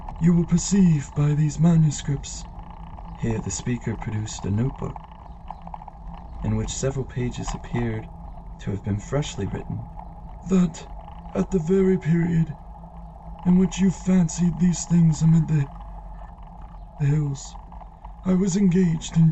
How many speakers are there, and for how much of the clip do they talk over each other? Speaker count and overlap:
1, no overlap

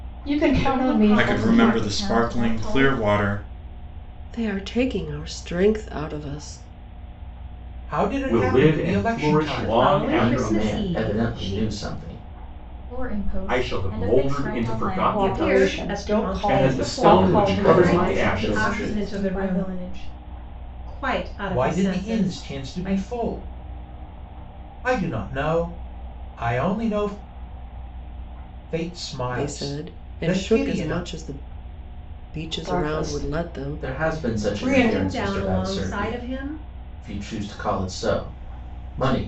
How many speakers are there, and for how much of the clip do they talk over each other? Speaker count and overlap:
8, about 48%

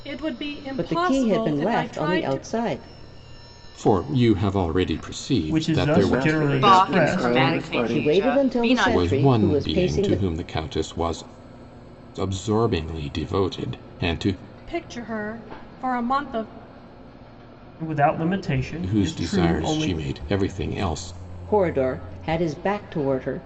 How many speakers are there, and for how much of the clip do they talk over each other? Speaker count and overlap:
6, about 33%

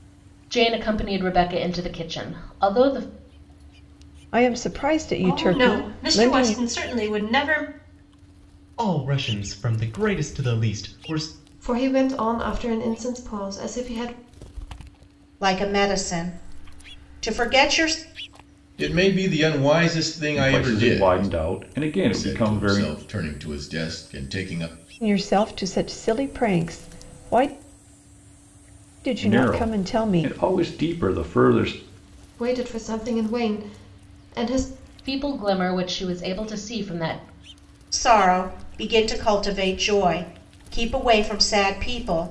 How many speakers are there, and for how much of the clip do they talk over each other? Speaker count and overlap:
8, about 10%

